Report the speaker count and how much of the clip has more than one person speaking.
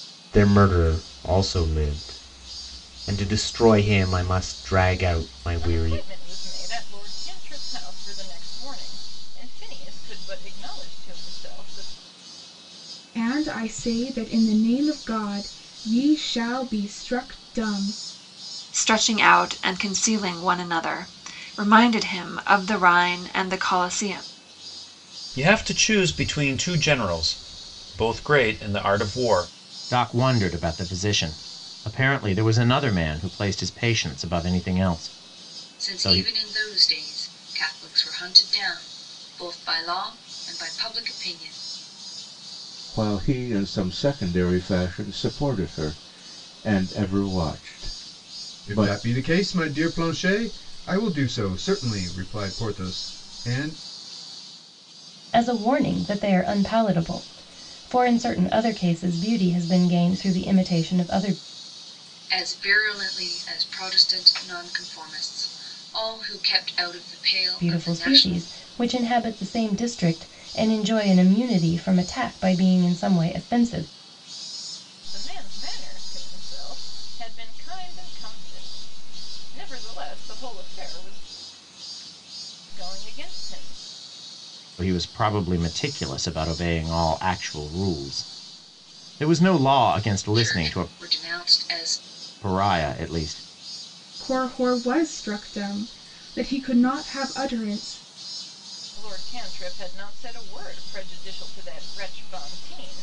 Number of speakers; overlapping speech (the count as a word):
ten, about 3%